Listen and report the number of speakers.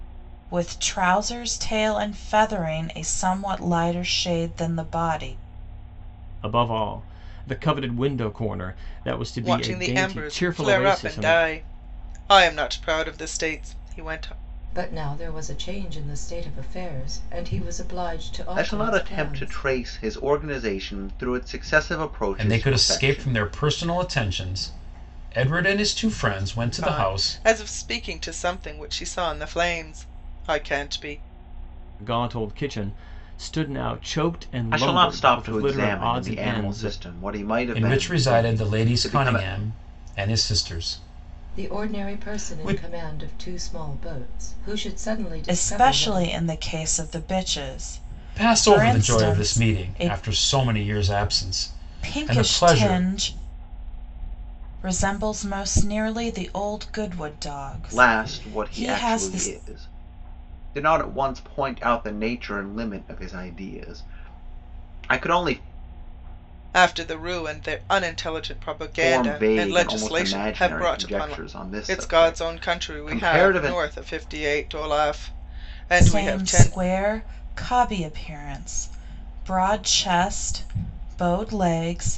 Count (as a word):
six